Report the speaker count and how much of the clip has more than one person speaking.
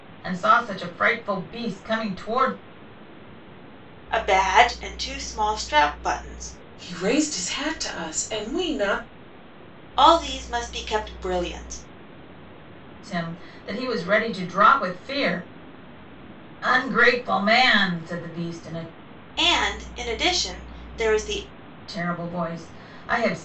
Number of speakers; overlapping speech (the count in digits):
3, no overlap